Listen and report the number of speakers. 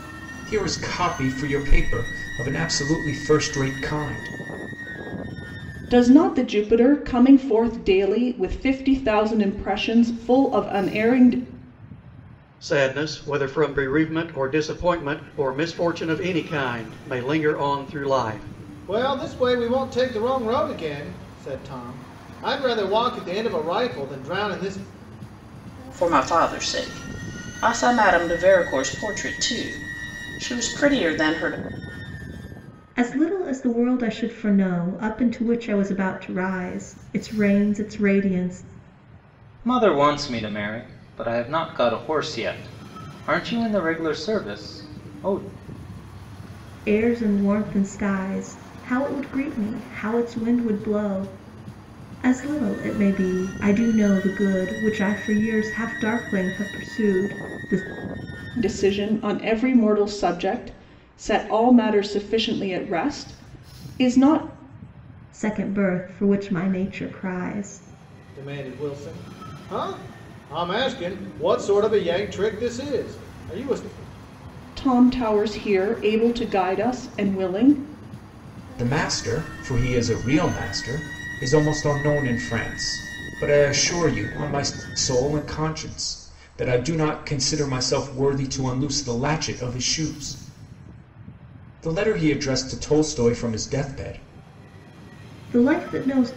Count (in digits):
7